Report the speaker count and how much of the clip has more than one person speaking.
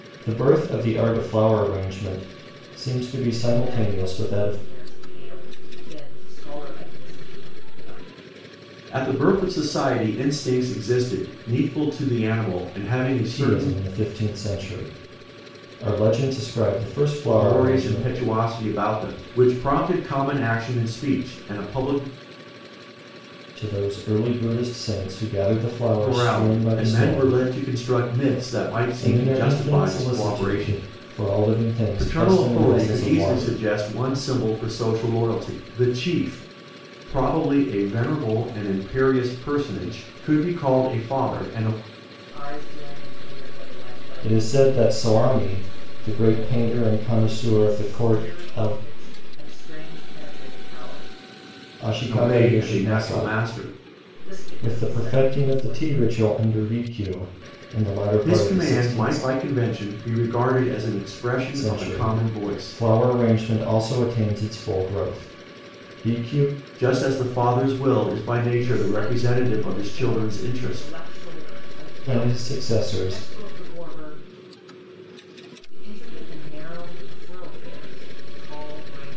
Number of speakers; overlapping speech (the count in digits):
3, about 26%